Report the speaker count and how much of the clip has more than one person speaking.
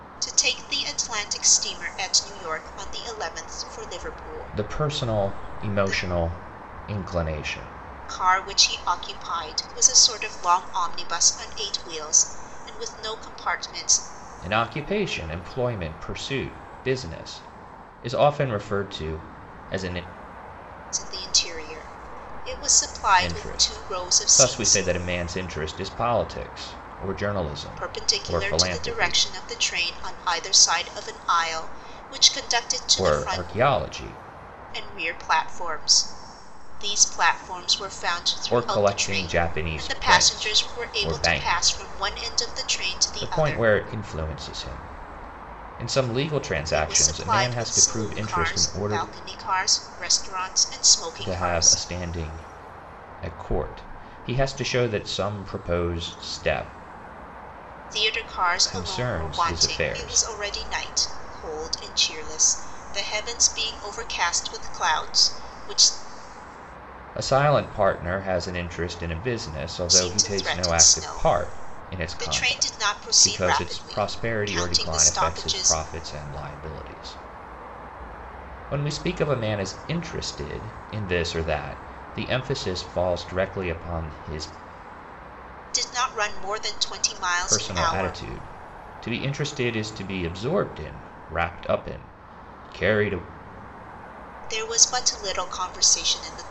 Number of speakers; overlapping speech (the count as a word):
two, about 21%